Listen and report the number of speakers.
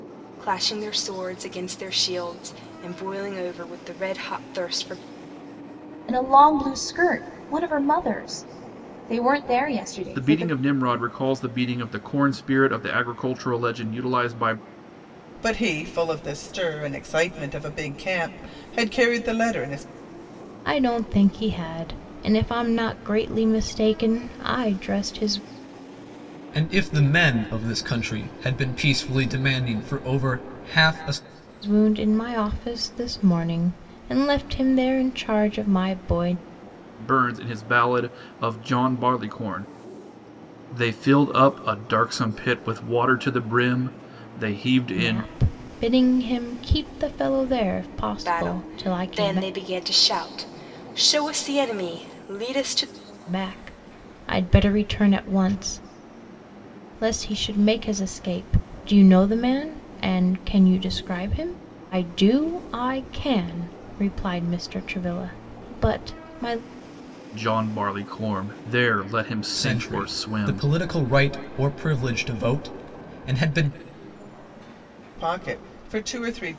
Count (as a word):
six